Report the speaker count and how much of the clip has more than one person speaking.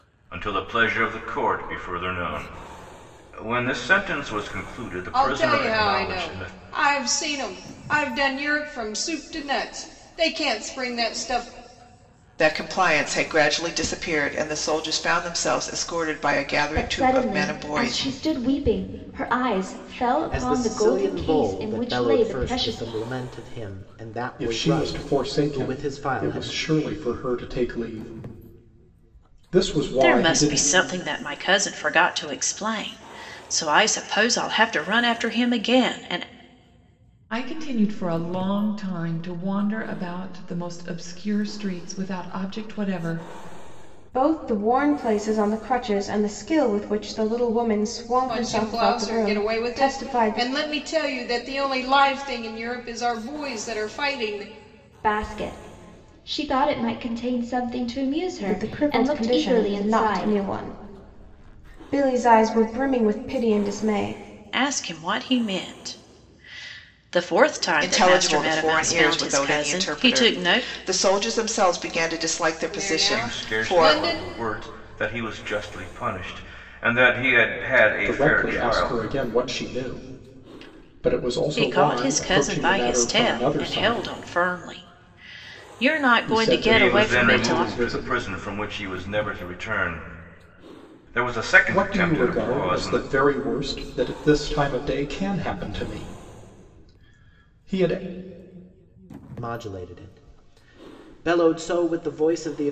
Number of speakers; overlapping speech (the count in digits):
9, about 23%